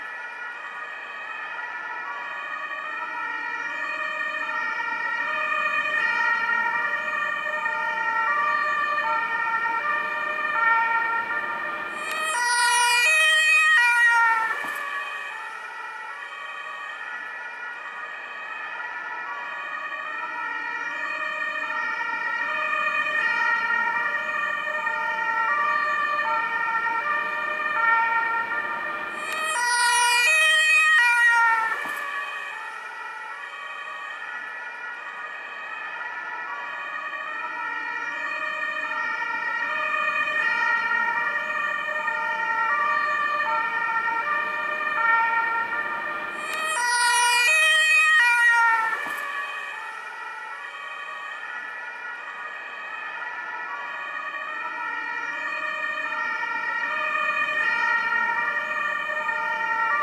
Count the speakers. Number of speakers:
0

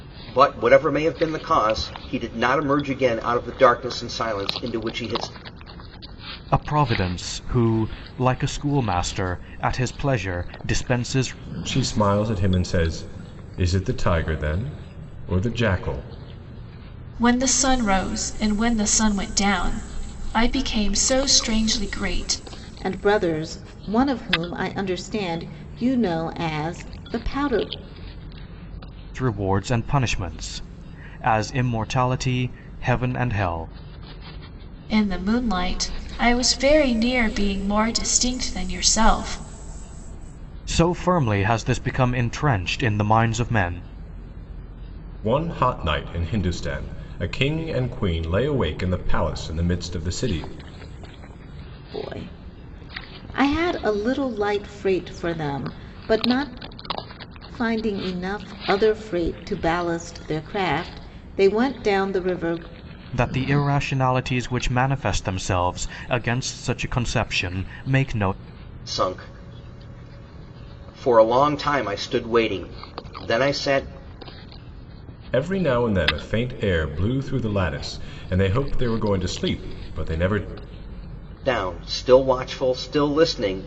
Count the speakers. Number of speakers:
5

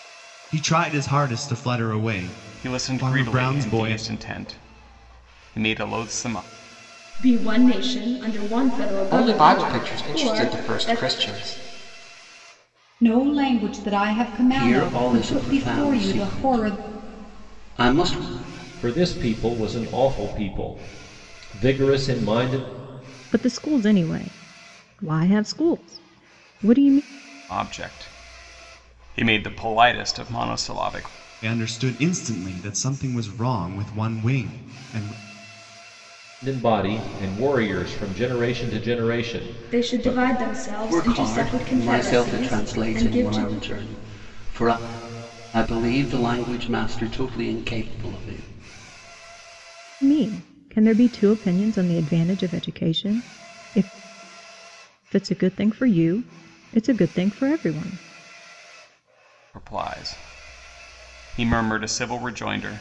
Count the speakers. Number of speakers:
8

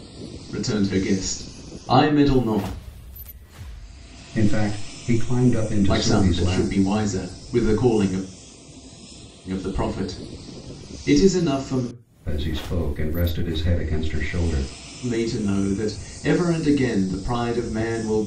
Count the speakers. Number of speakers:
2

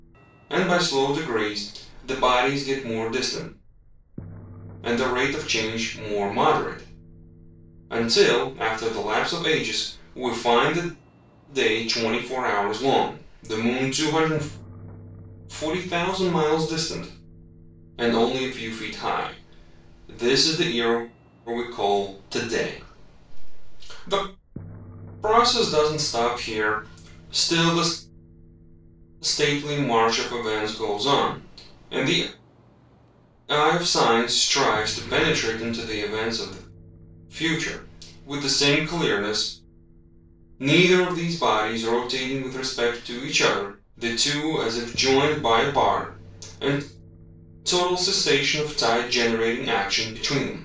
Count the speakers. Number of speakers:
1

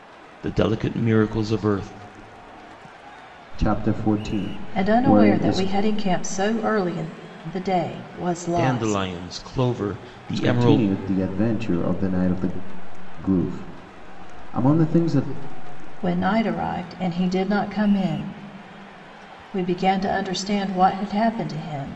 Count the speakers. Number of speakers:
3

